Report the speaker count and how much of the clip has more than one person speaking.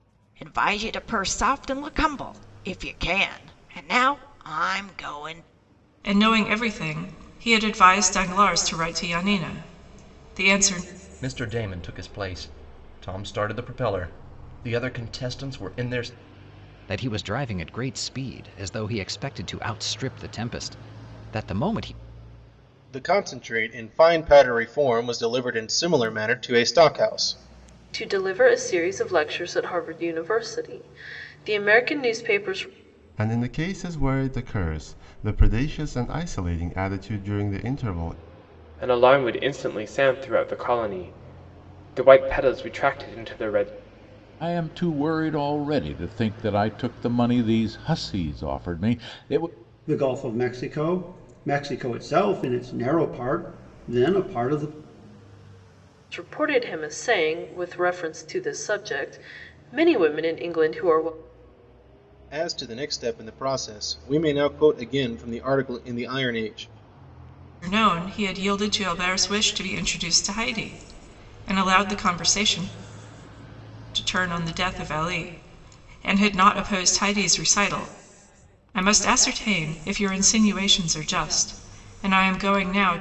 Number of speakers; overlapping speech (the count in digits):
10, no overlap